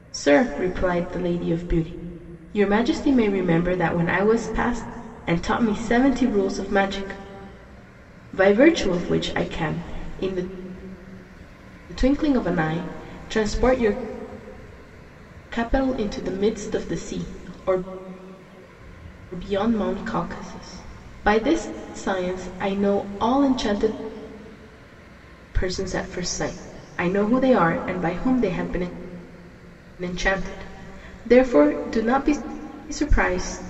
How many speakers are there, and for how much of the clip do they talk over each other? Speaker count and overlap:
1, no overlap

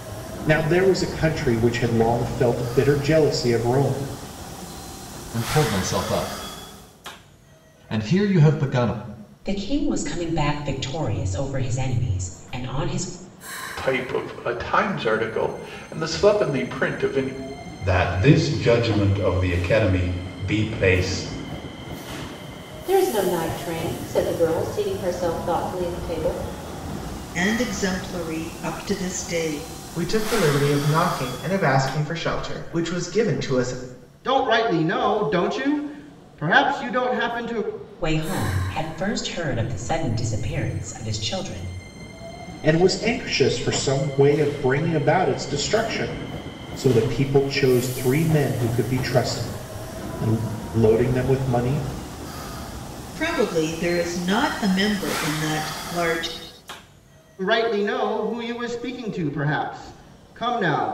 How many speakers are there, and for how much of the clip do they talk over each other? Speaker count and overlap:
9, no overlap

